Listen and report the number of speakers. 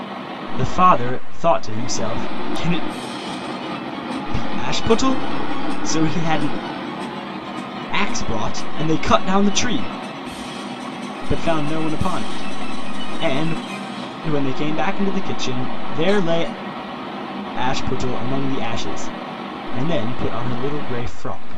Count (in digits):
1